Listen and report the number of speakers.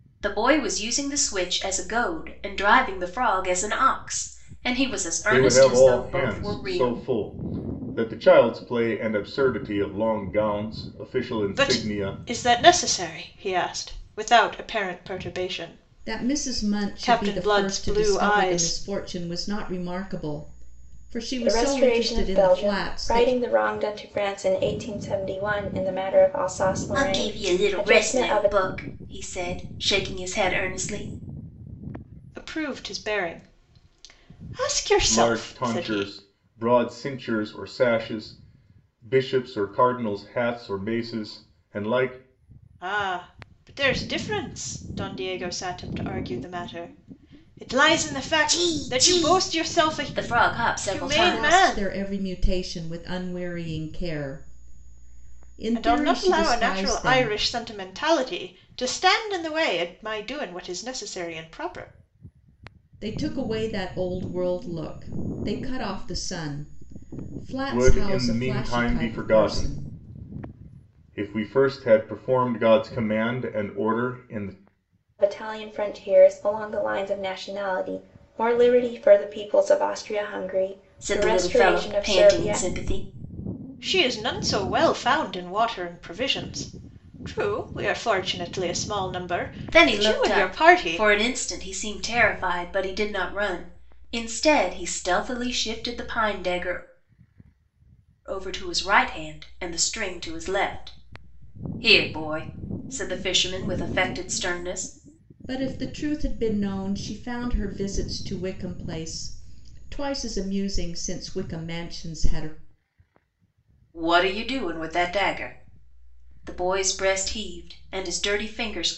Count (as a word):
five